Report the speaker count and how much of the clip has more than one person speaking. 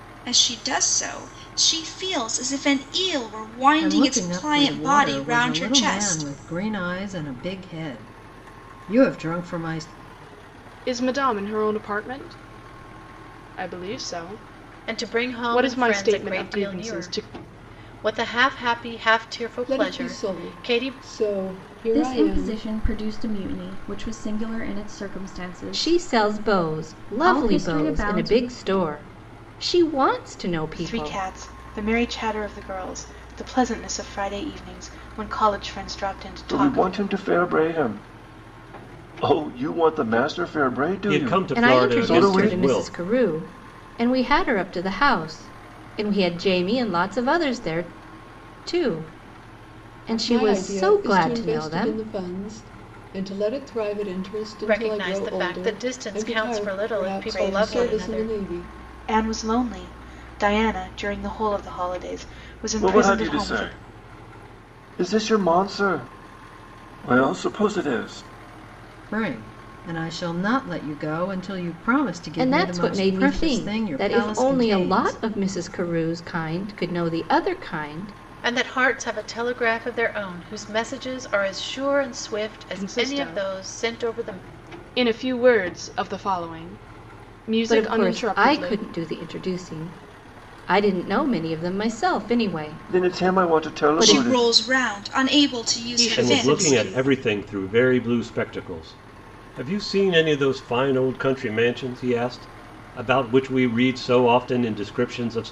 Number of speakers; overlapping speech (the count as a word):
ten, about 27%